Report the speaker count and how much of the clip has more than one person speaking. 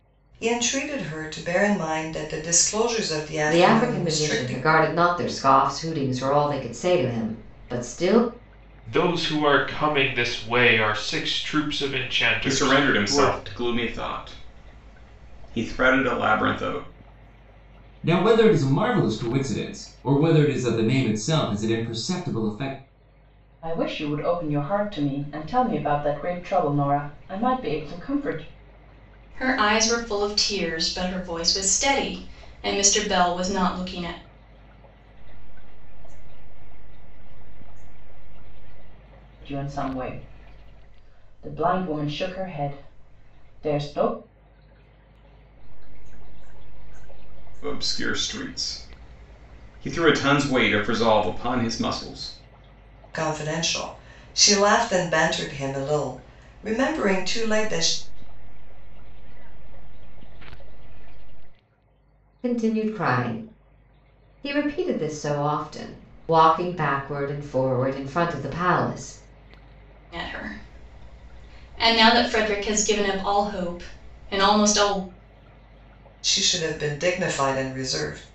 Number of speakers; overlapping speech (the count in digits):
8, about 5%